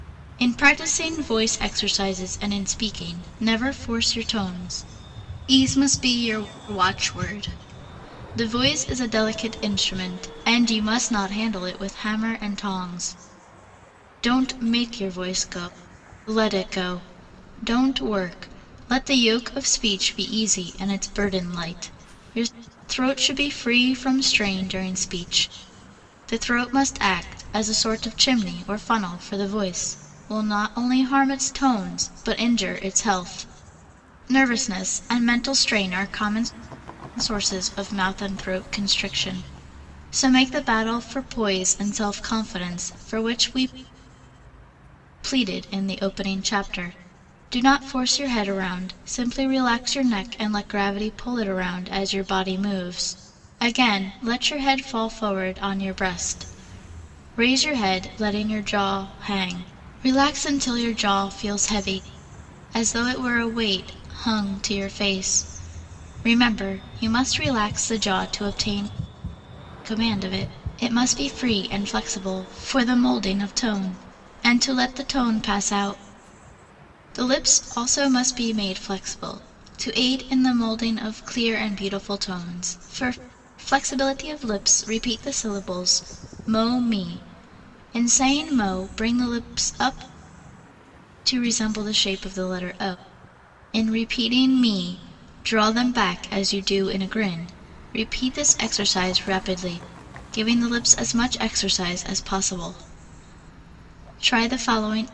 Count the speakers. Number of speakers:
one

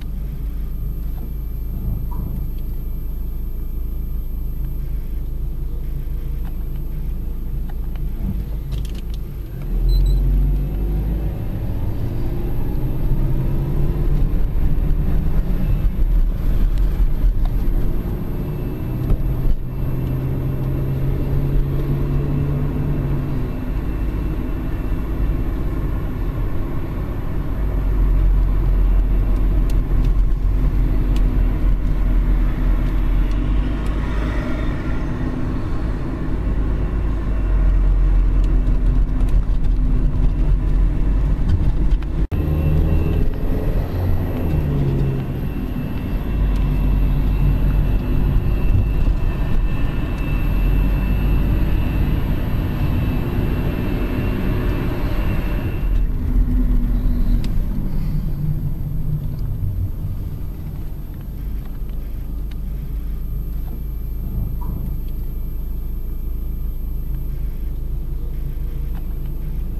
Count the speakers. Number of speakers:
zero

